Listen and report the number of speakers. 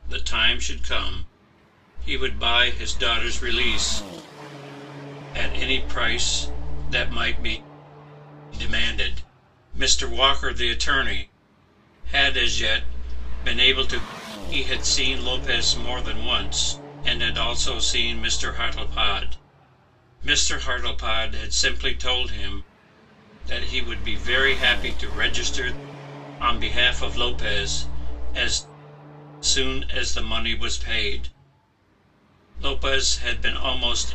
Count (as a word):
one